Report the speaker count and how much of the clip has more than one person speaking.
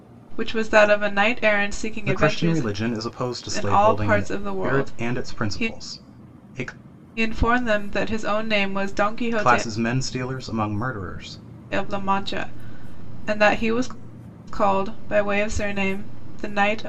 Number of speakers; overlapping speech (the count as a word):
two, about 19%